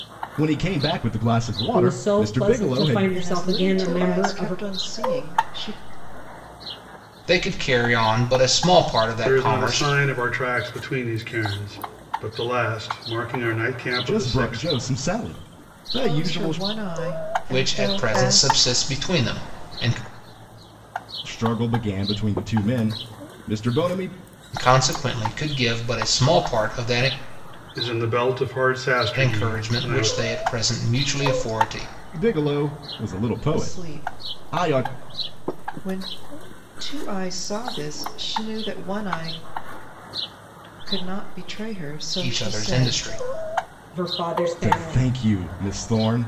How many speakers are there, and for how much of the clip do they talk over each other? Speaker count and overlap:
five, about 22%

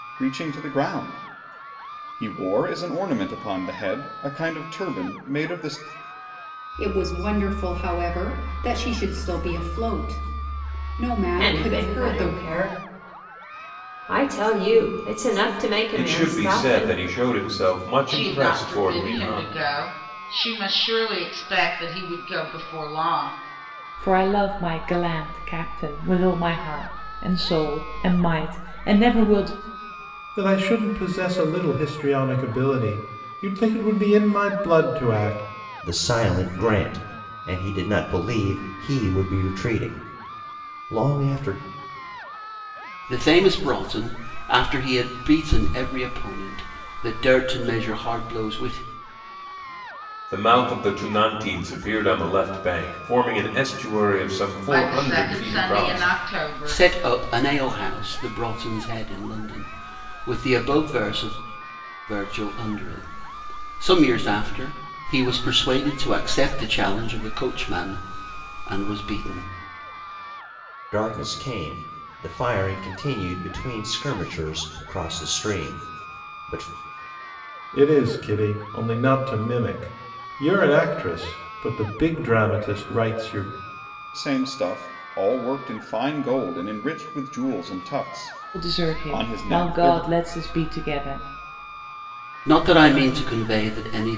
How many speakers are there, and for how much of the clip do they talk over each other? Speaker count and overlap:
nine, about 8%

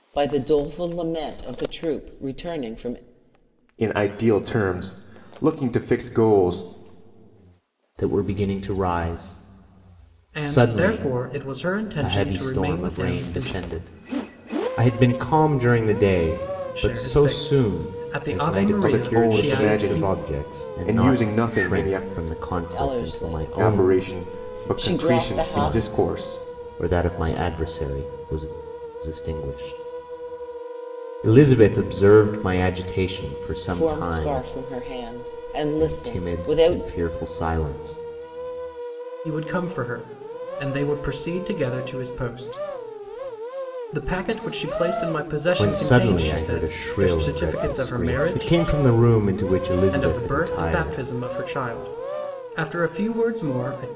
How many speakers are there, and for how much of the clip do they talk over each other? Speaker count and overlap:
four, about 31%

